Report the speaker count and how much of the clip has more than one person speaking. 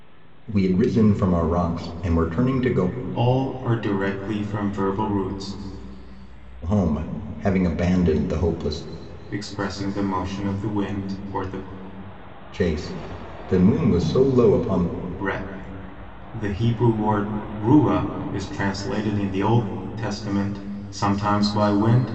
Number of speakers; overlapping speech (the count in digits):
2, no overlap